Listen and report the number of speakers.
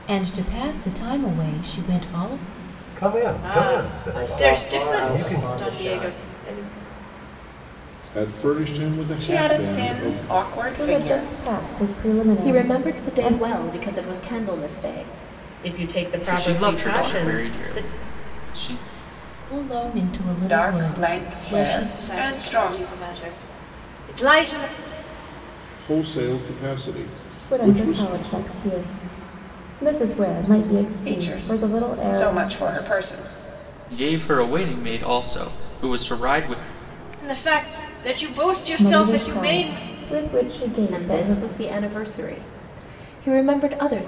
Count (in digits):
10